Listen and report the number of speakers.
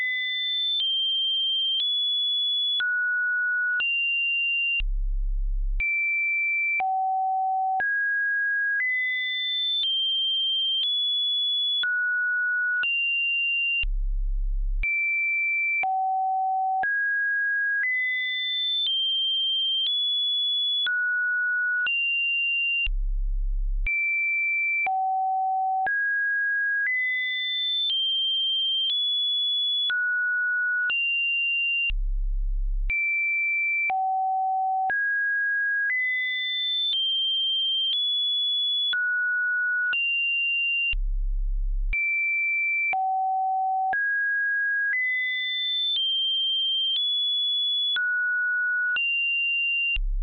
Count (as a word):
zero